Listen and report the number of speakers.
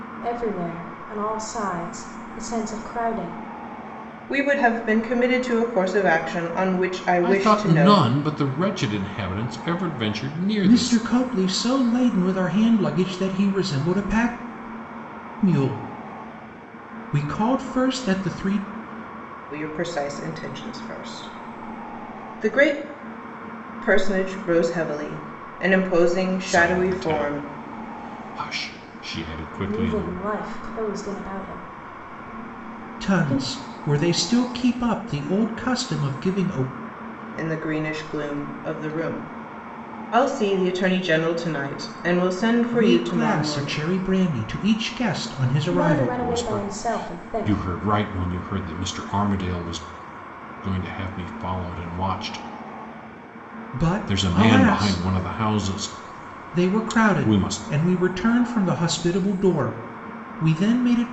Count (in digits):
4